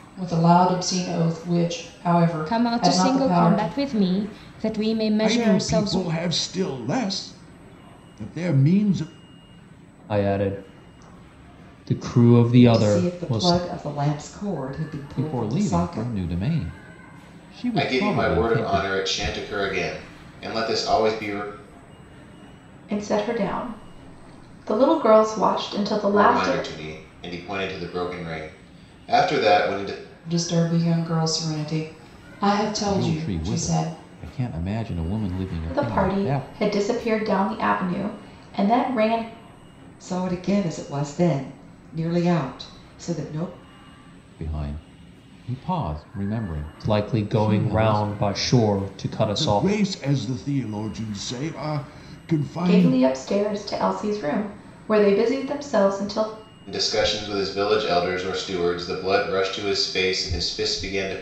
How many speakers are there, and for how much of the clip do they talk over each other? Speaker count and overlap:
eight, about 16%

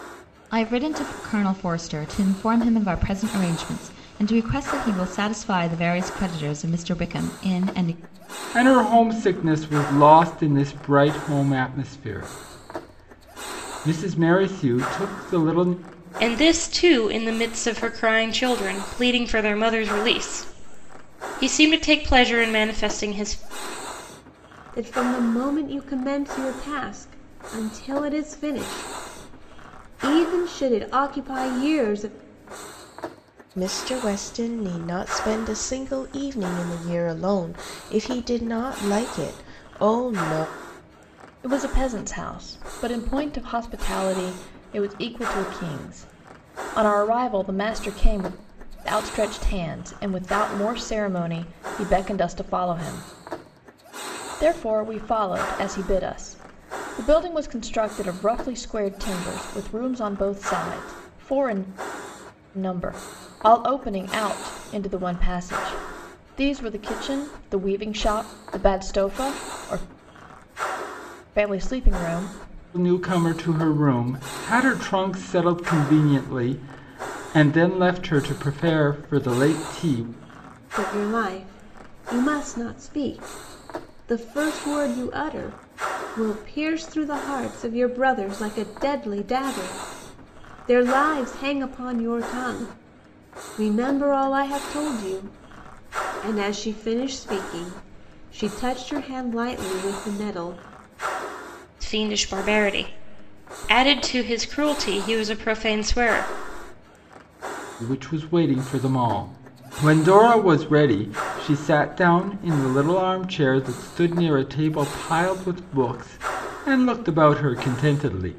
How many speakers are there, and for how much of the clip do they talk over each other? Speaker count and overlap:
six, no overlap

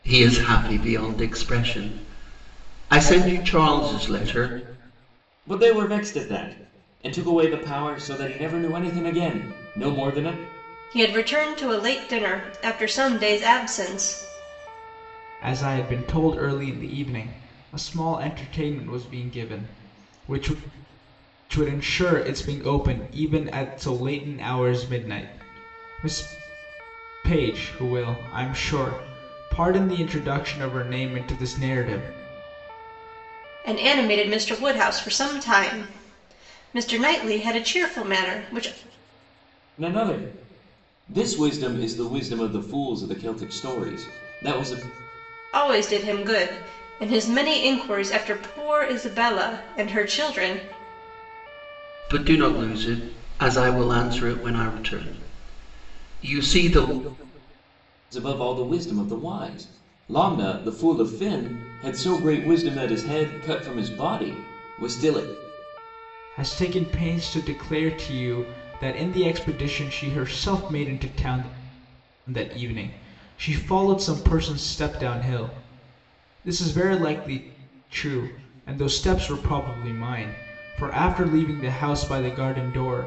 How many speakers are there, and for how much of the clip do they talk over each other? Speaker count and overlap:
four, no overlap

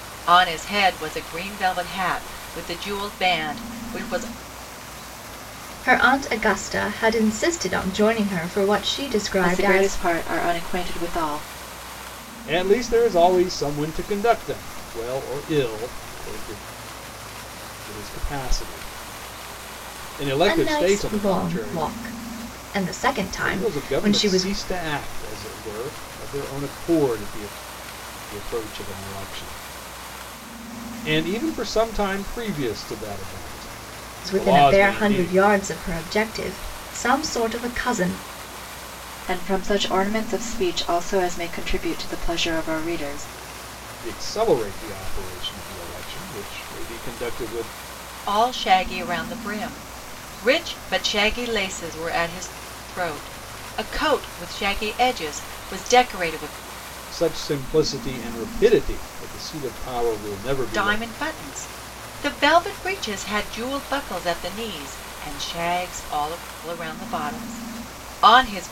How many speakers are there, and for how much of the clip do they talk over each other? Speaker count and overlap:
four, about 7%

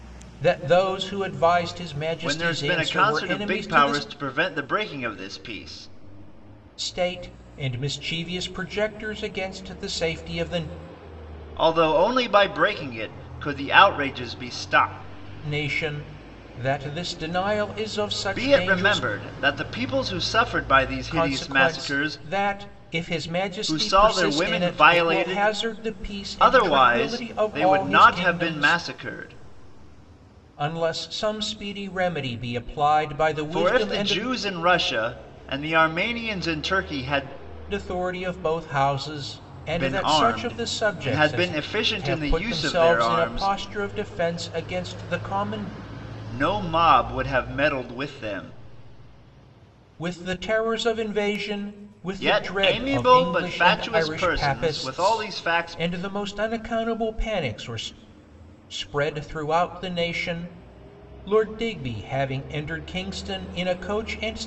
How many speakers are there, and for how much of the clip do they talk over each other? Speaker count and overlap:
two, about 25%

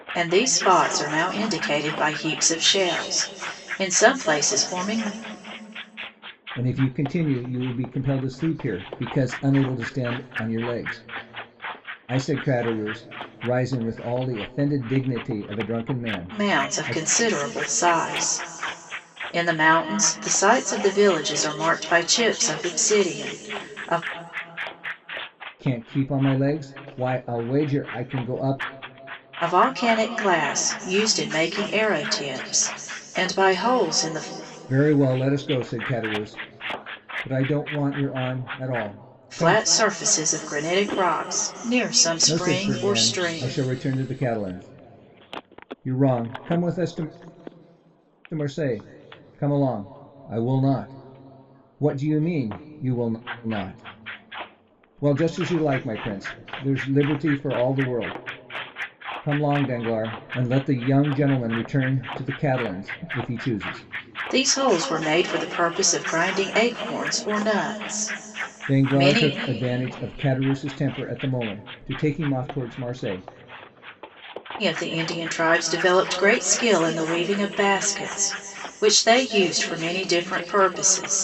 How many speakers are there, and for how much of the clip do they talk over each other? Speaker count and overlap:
two, about 4%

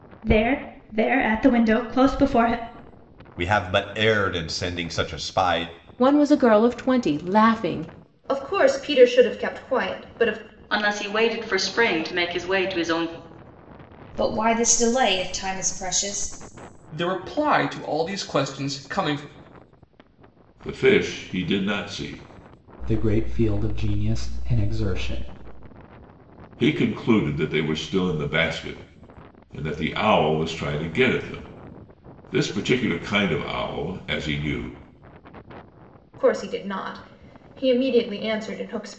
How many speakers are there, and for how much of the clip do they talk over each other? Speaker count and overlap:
nine, no overlap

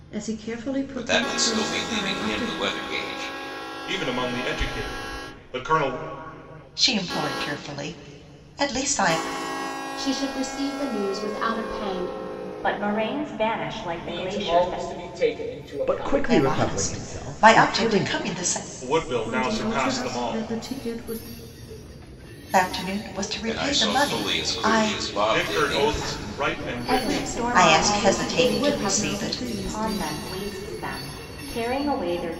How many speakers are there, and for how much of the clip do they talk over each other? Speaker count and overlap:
eight, about 39%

